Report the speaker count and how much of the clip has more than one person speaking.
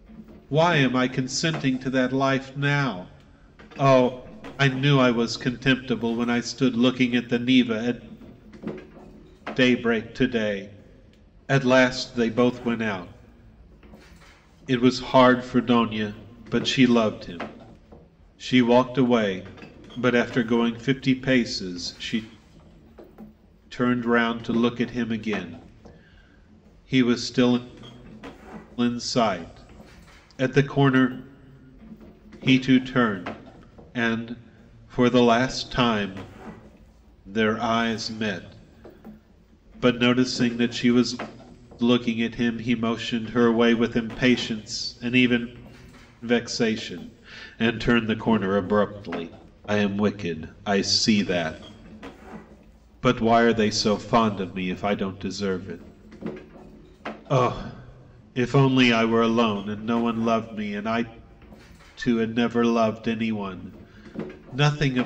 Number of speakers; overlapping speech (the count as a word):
one, no overlap